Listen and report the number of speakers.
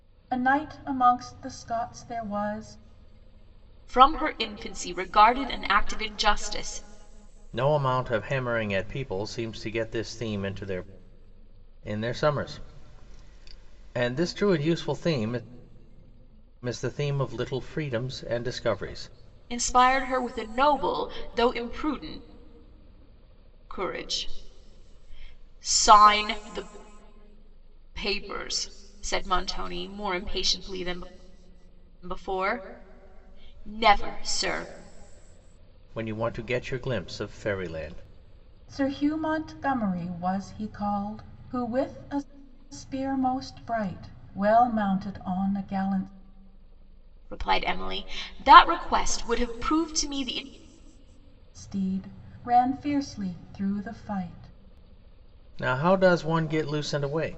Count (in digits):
3